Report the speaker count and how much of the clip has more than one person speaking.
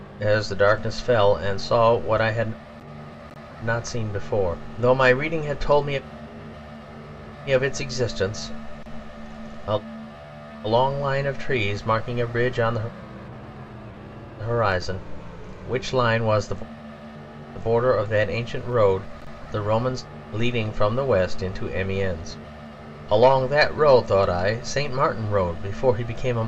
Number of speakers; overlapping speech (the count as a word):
one, no overlap